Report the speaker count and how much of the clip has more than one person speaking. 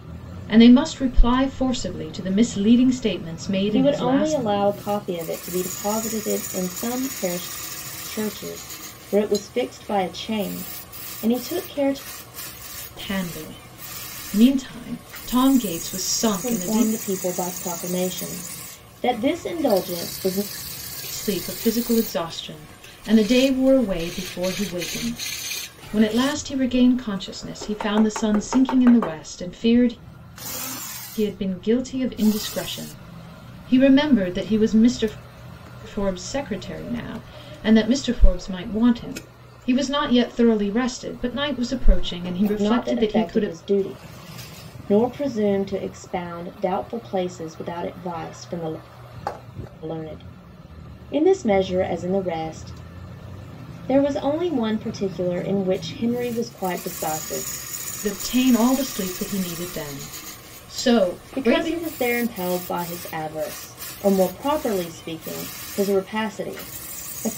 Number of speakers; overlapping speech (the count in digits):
2, about 4%